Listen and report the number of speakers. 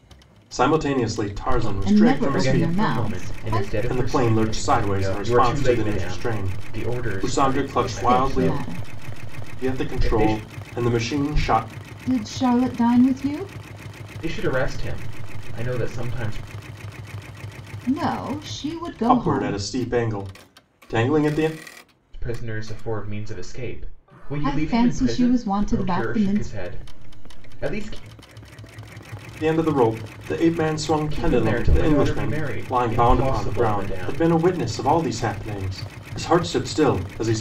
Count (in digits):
3